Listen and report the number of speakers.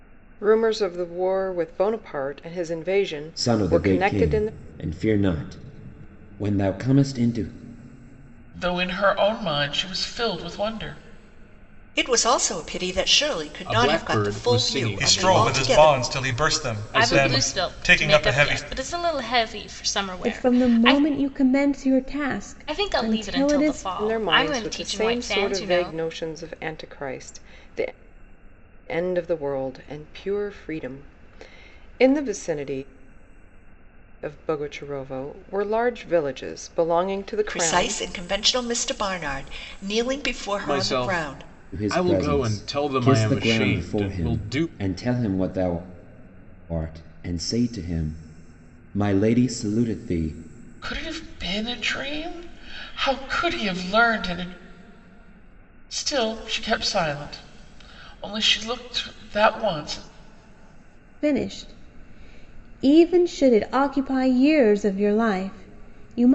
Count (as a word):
eight